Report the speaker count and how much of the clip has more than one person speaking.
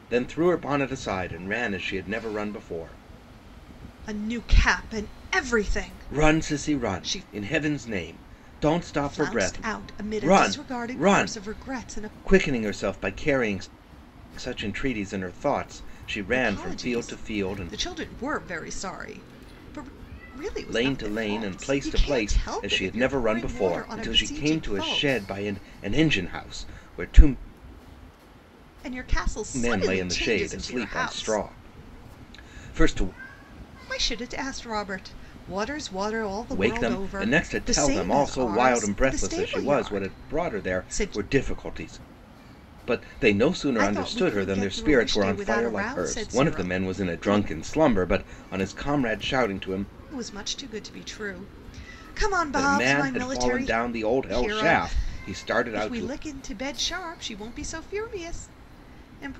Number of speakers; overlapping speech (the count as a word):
two, about 38%